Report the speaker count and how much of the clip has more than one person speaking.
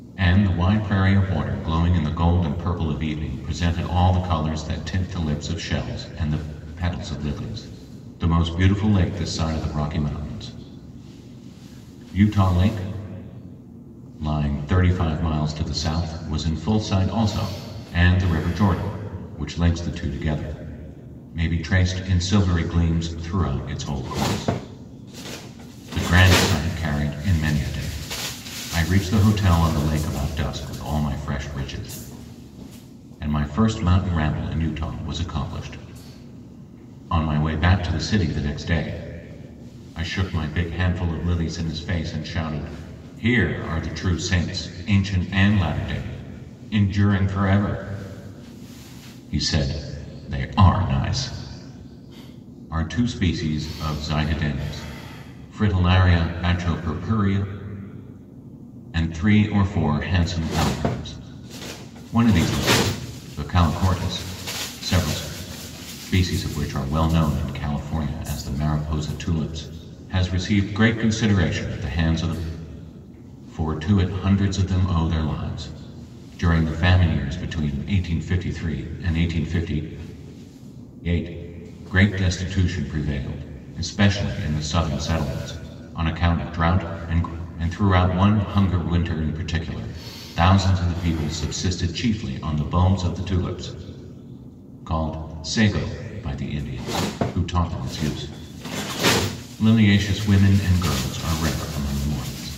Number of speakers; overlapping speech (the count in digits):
1, no overlap